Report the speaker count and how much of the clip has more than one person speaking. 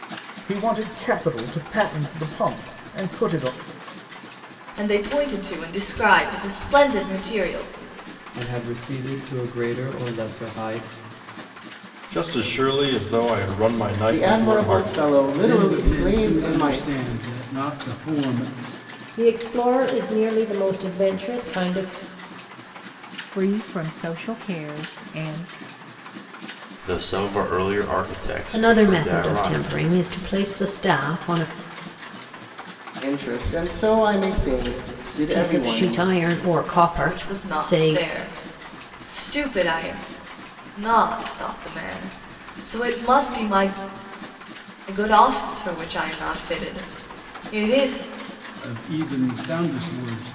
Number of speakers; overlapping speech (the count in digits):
10, about 11%